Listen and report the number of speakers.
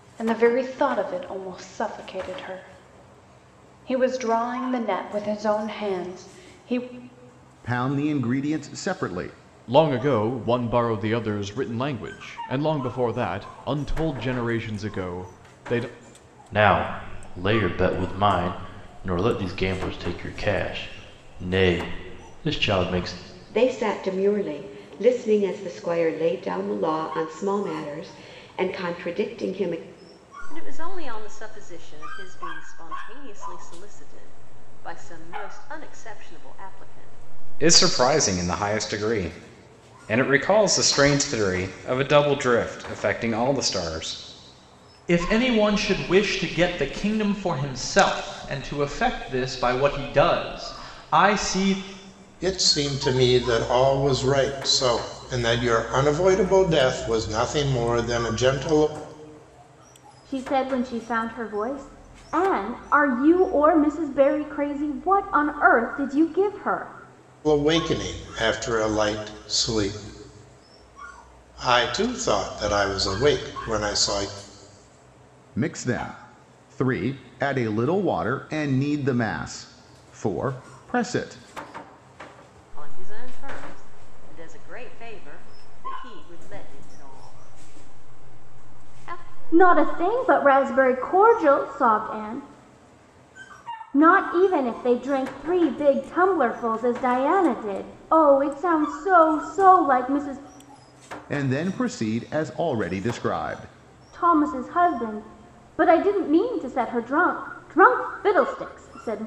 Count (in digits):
10